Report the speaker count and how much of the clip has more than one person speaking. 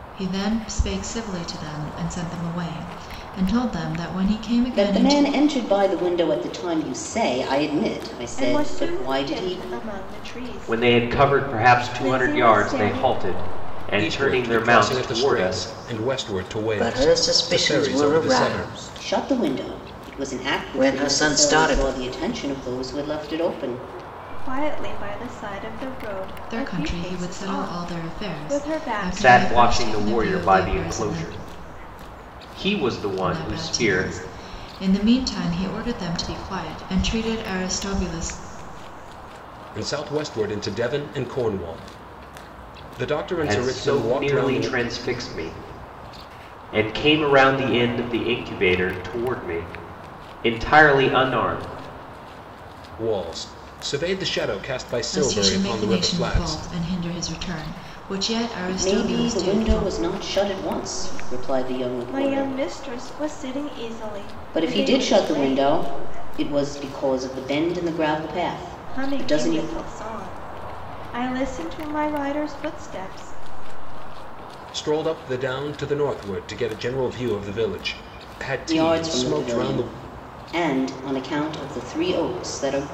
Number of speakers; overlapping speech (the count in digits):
6, about 31%